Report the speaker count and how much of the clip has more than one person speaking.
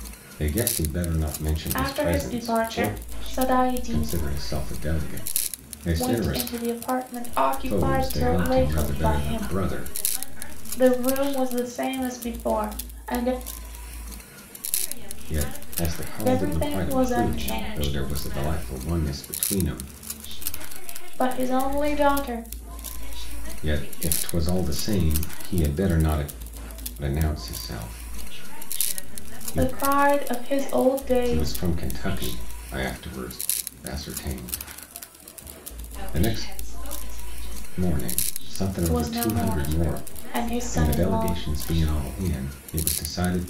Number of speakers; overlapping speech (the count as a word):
three, about 55%